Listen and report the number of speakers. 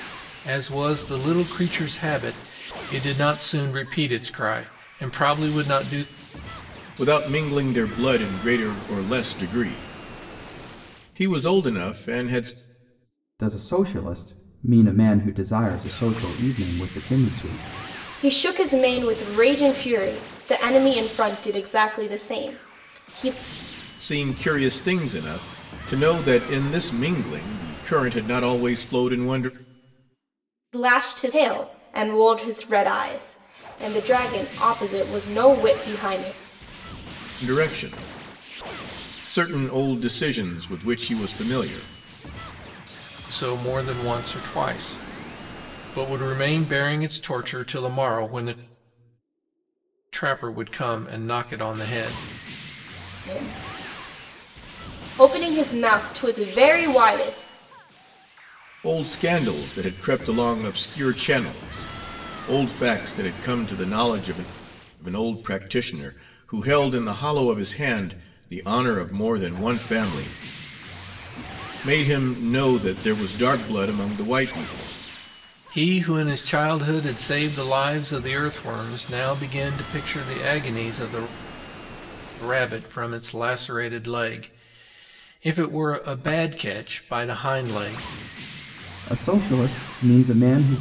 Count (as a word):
four